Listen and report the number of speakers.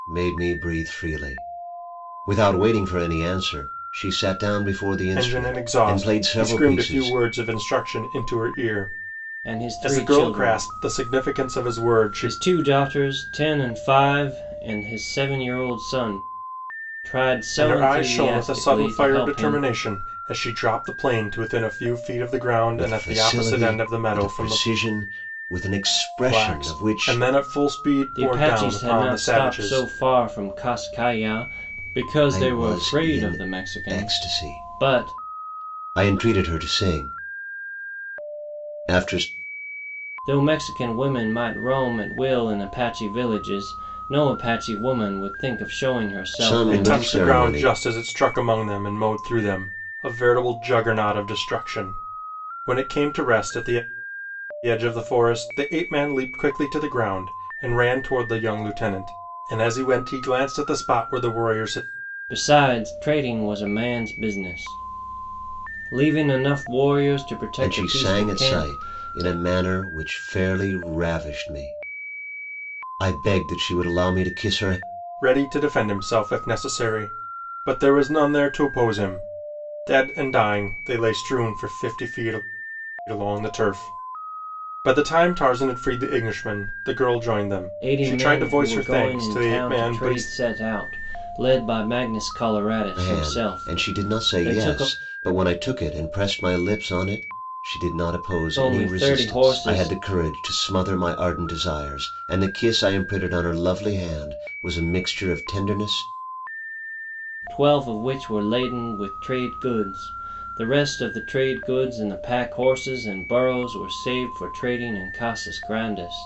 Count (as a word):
three